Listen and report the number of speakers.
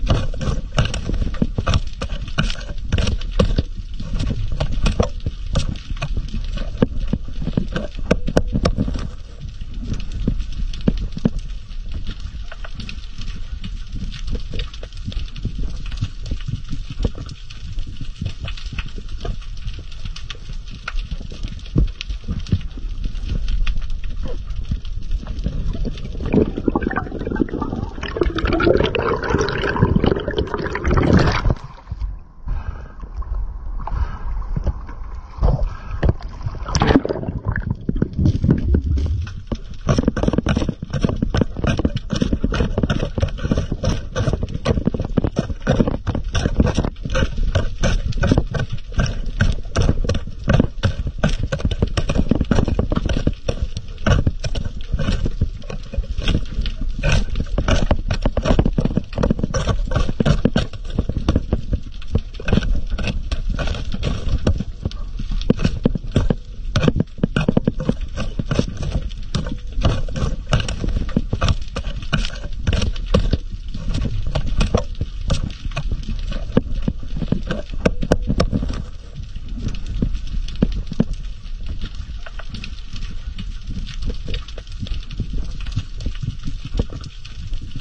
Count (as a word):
zero